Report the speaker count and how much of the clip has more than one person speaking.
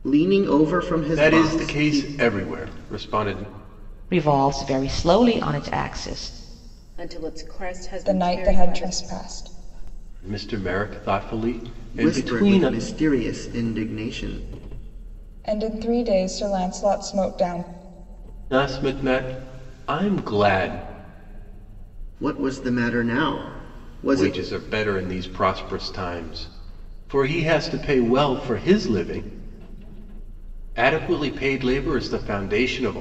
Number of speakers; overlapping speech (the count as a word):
five, about 9%